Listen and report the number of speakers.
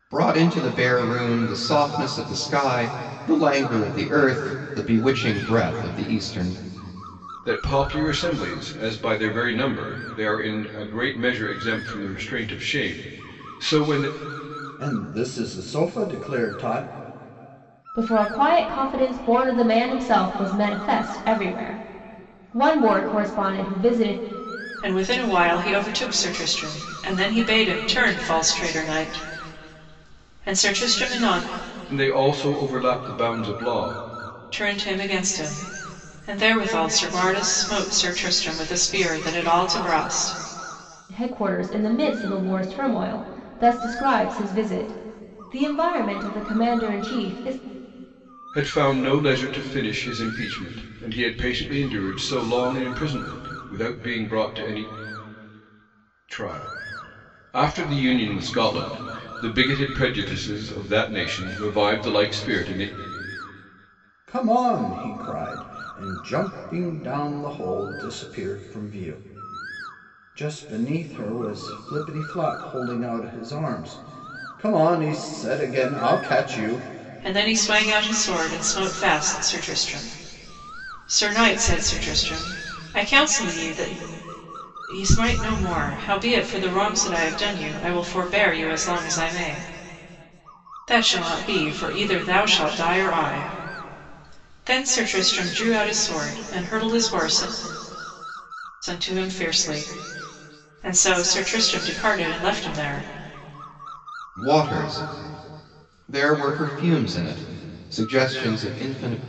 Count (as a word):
five